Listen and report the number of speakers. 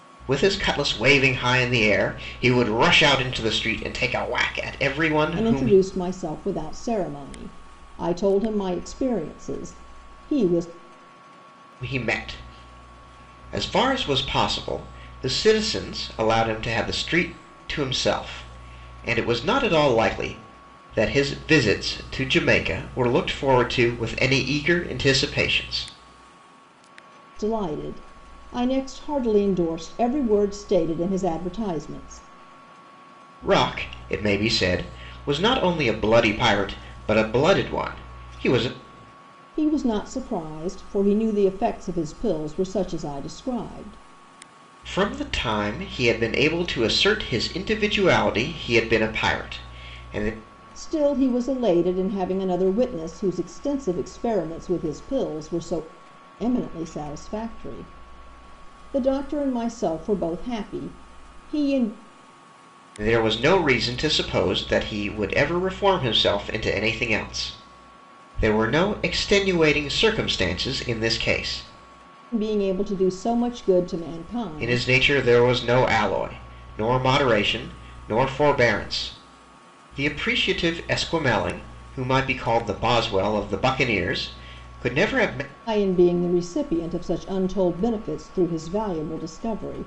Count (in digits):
2